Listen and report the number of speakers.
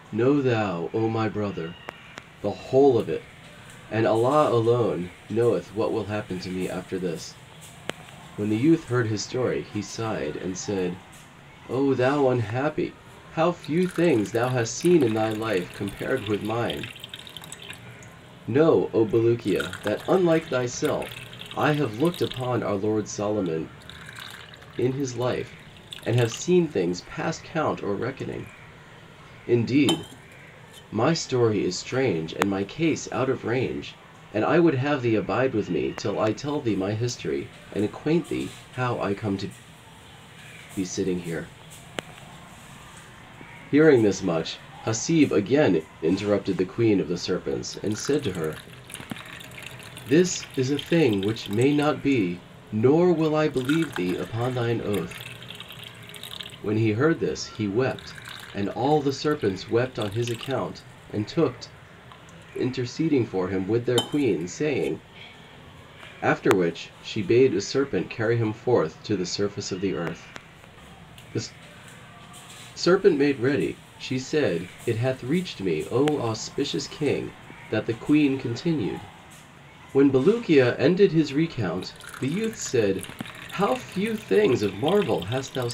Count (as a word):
one